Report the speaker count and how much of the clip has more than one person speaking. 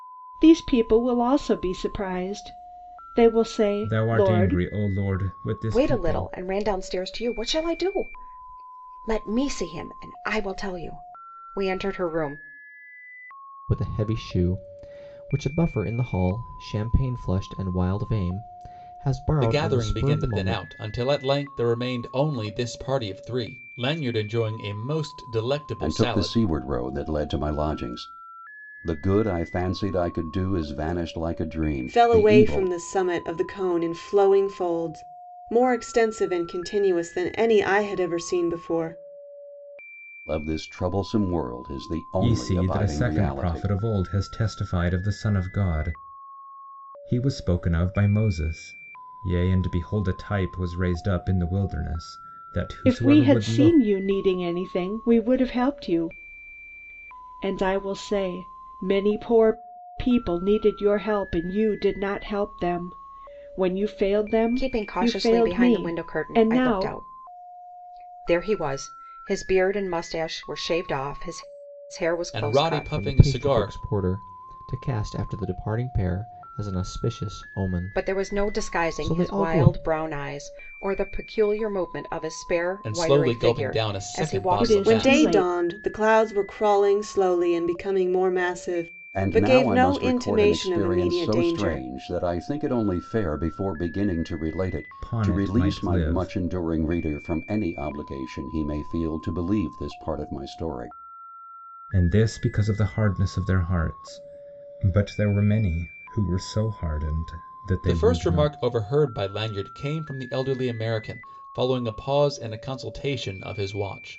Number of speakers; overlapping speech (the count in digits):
7, about 18%